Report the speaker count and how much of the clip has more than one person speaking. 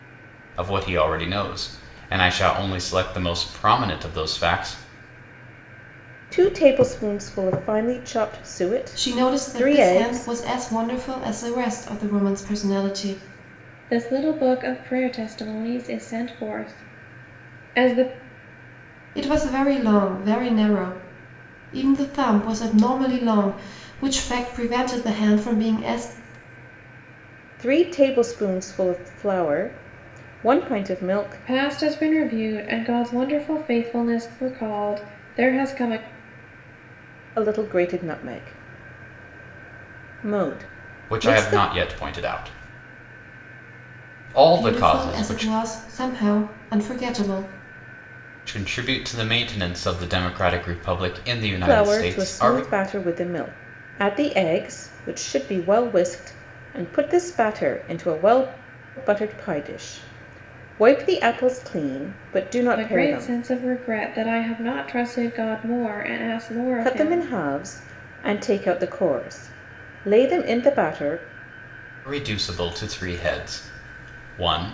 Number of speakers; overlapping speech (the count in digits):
4, about 8%